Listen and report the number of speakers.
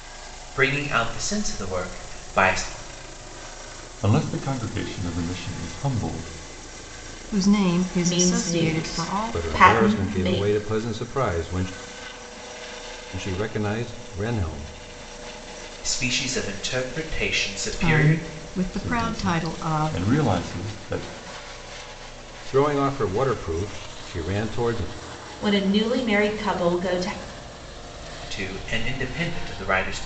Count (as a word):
five